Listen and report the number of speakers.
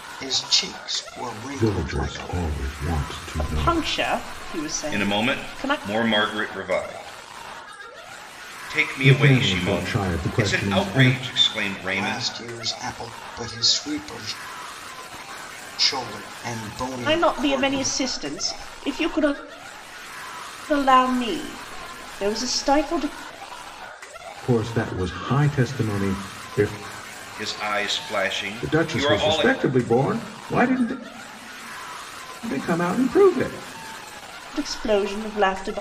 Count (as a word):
four